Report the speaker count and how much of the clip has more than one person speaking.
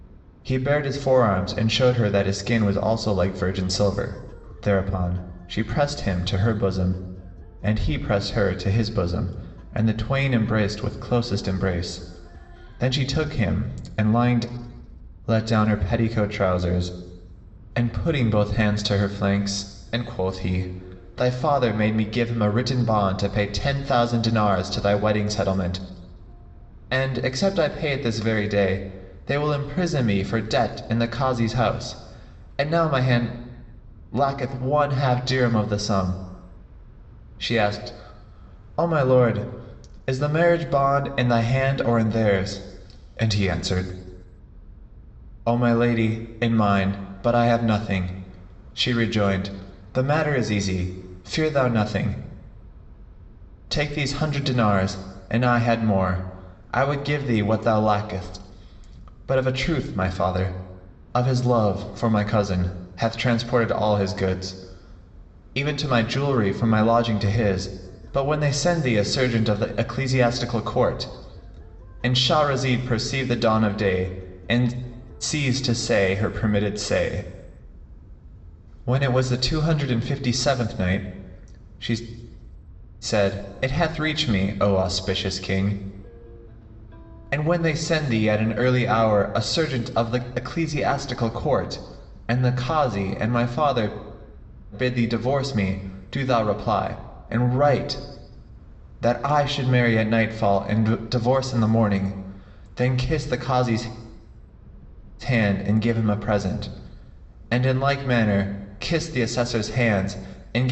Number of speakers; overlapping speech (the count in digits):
1, no overlap